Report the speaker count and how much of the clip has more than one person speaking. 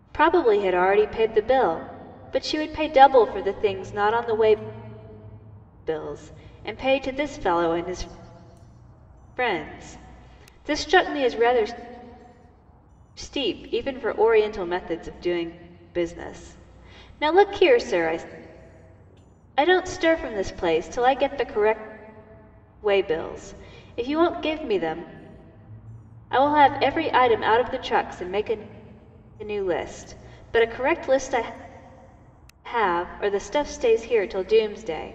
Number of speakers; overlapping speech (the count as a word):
one, no overlap